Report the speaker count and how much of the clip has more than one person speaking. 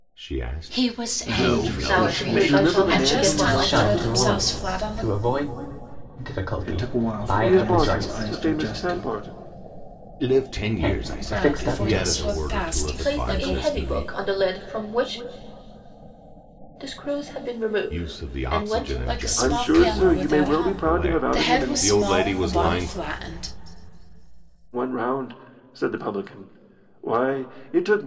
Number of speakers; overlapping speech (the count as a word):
seven, about 54%